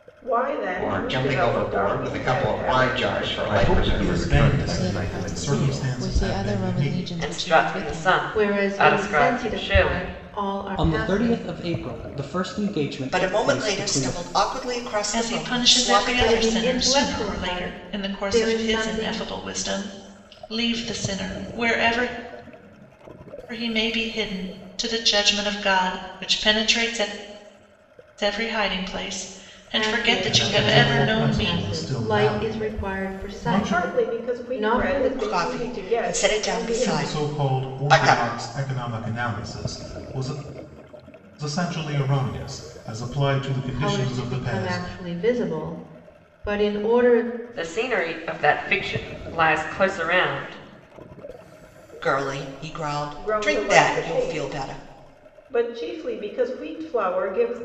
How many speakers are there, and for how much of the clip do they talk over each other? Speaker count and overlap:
10, about 46%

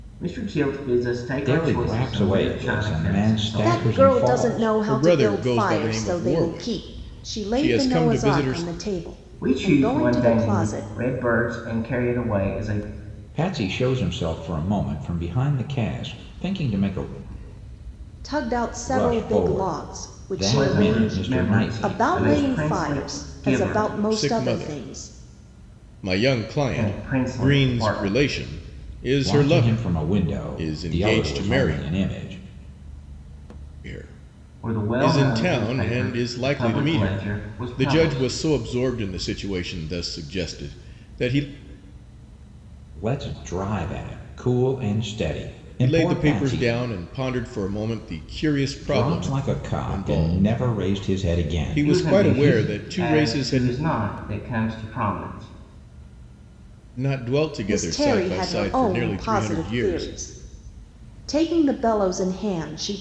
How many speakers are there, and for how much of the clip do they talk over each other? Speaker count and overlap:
4, about 47%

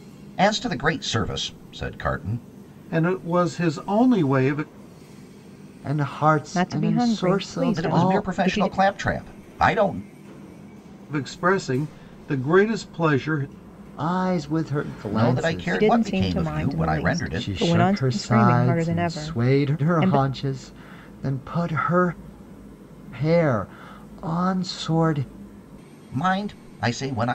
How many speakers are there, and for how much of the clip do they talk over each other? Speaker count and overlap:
4, about 26%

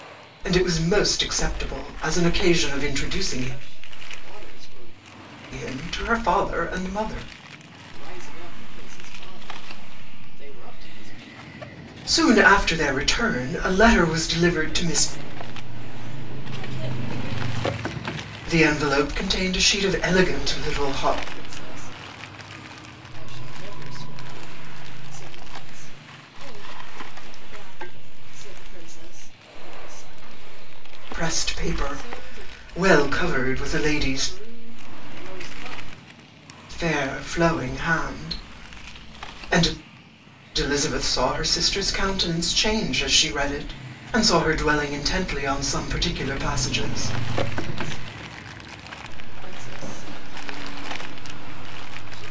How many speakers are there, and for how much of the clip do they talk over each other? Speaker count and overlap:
2, about 12%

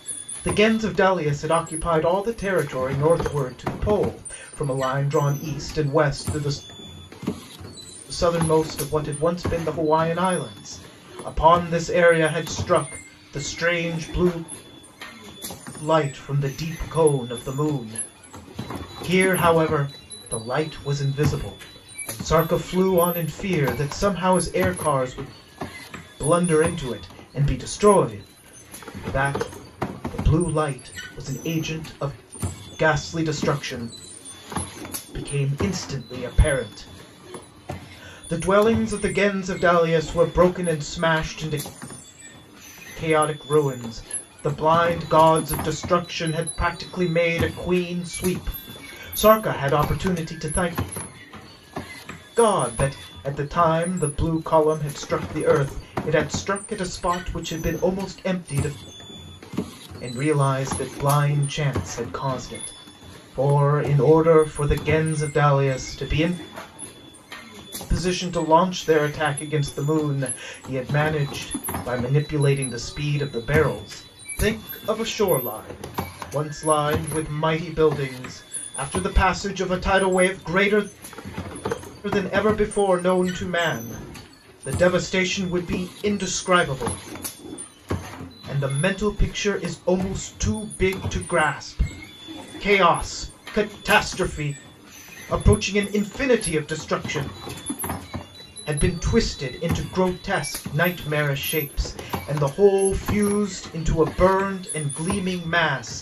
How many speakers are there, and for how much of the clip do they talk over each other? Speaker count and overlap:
1, no overlap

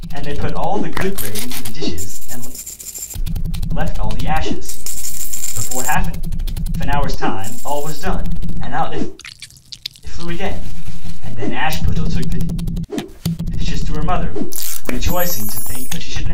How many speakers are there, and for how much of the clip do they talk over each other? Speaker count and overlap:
1, no overlap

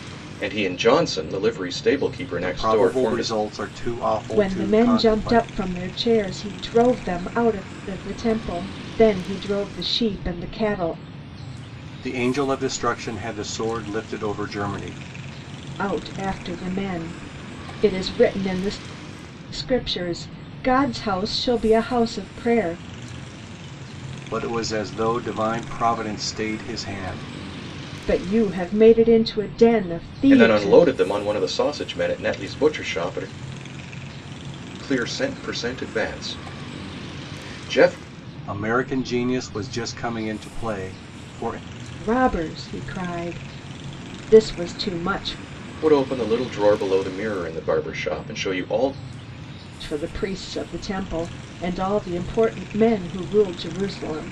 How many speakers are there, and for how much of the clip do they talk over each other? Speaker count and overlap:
3, about 5%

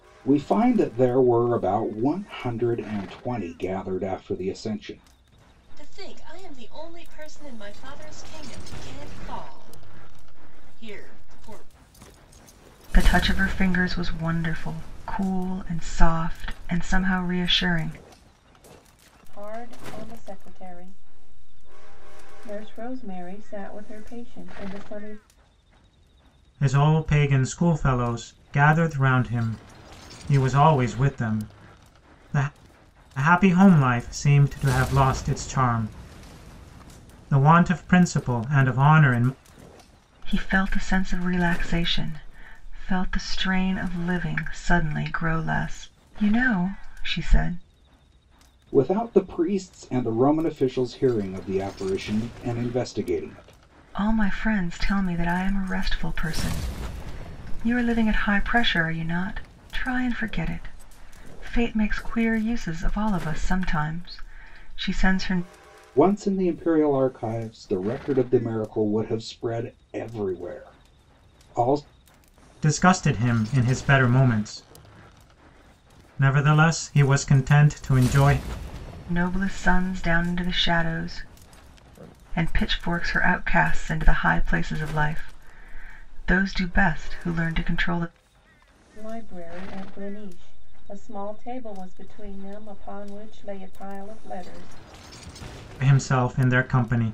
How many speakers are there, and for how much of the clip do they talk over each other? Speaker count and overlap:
5, no overlap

